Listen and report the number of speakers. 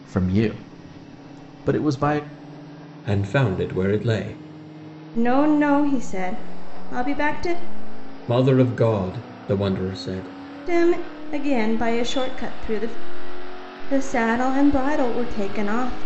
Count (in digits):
3